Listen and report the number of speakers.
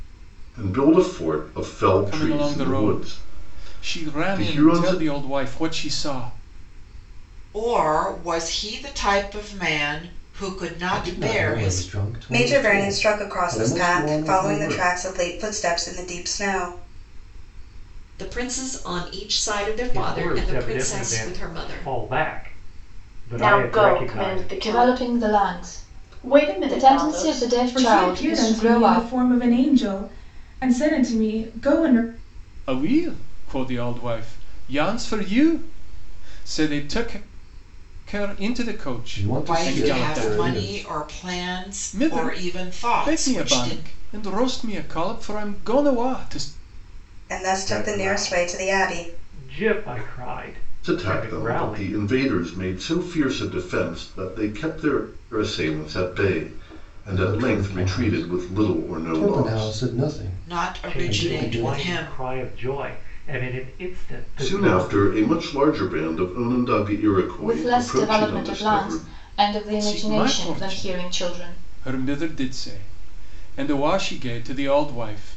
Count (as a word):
ten